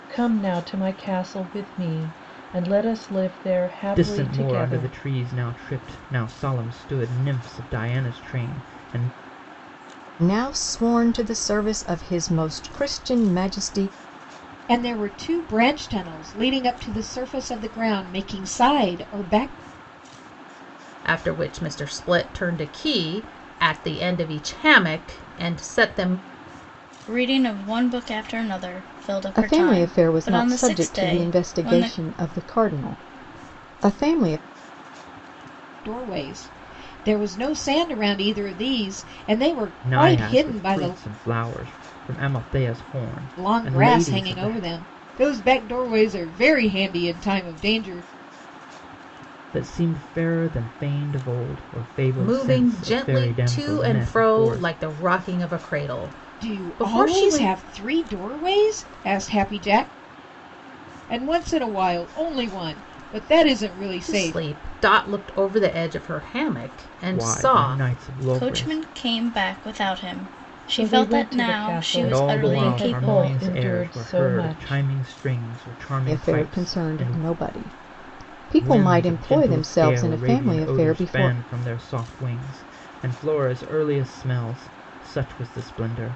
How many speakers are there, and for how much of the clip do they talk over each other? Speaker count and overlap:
6, about 23%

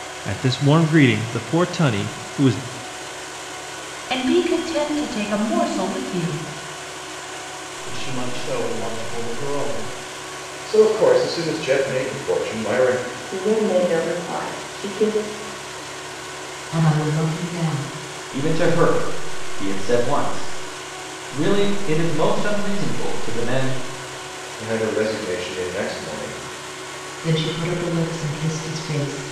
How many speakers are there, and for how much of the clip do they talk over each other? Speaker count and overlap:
7, no overlap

